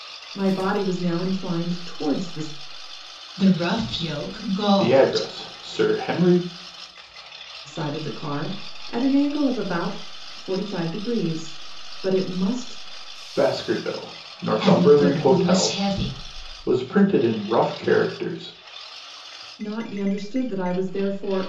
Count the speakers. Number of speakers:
3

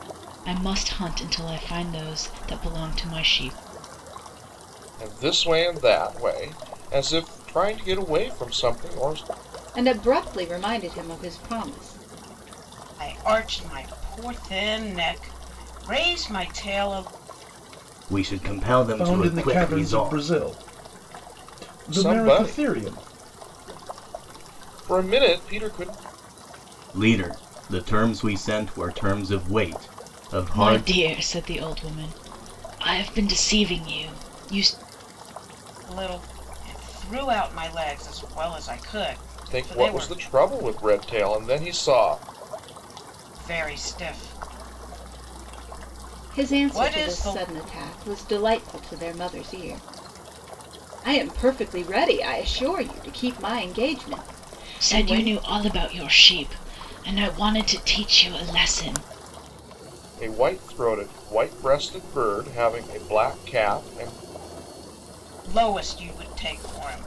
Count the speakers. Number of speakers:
6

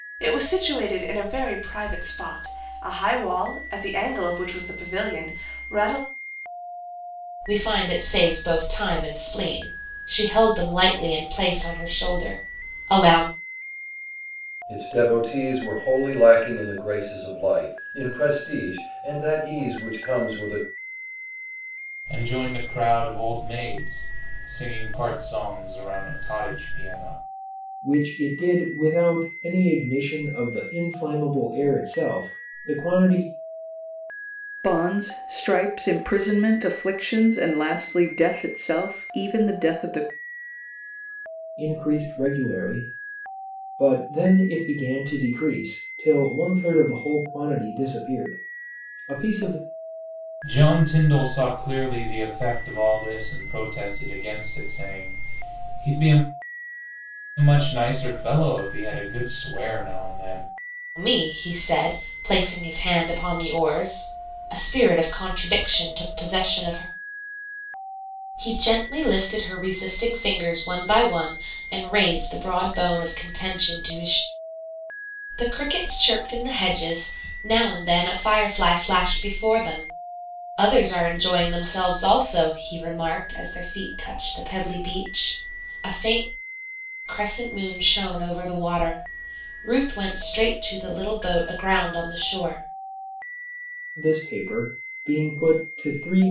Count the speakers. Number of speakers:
6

